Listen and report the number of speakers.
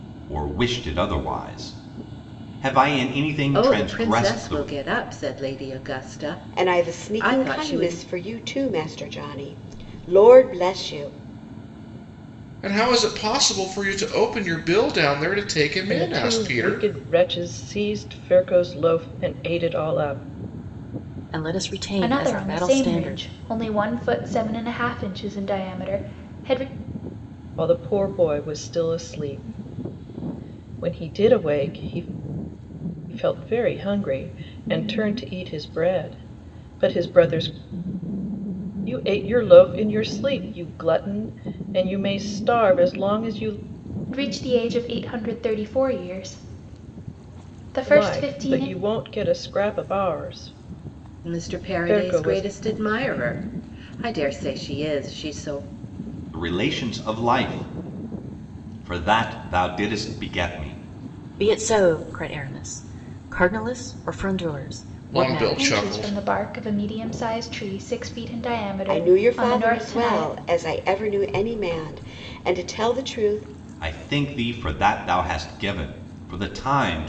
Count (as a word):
seven